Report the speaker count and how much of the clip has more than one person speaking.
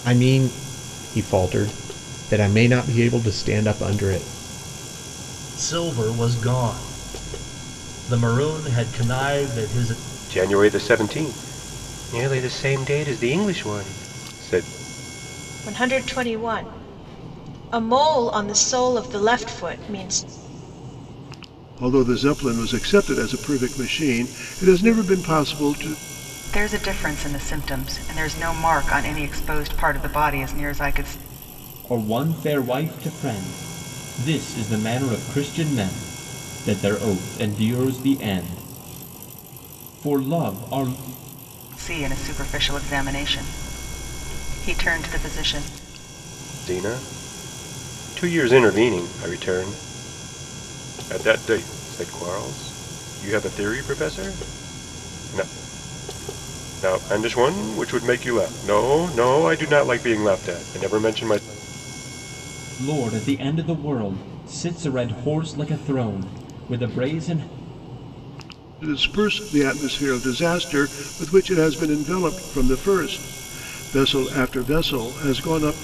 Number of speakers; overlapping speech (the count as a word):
seven, no overlap